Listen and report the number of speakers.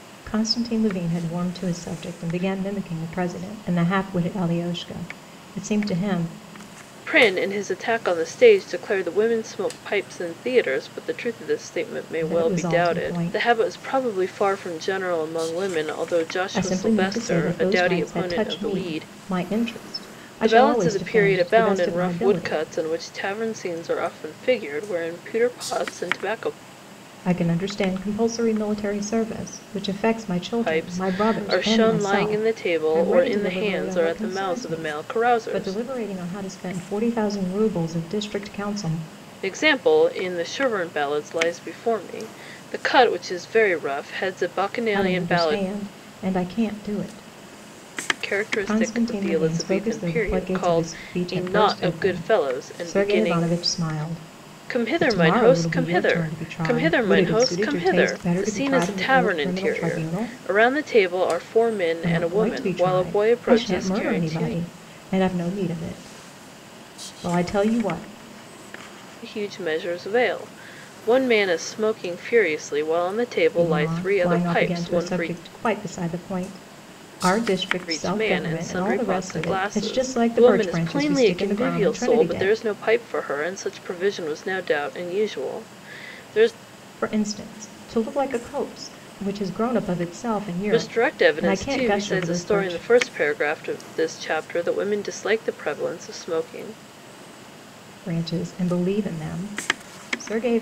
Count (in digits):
2